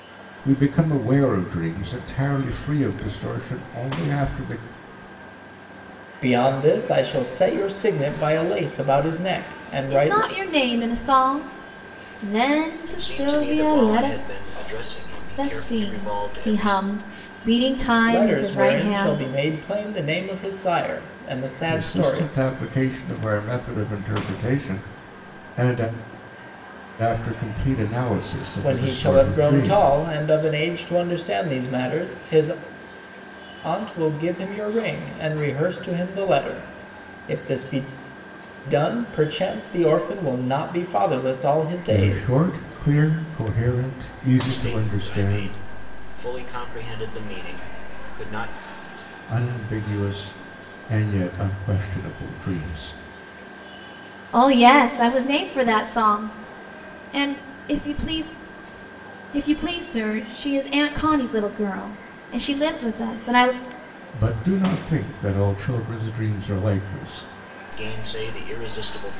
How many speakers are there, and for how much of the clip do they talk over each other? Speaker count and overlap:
4, about 11%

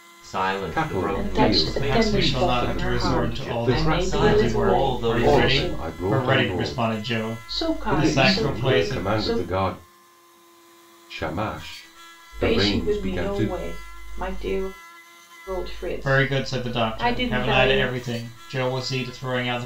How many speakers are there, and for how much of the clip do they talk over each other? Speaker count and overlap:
4, about 57%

